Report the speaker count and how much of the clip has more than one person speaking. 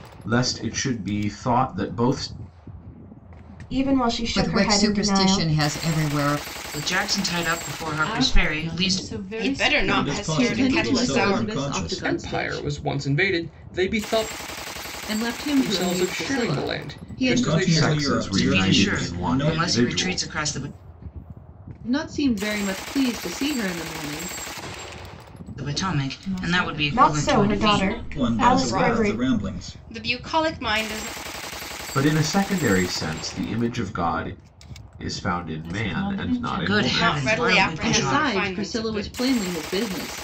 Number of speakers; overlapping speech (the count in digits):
9, about 43%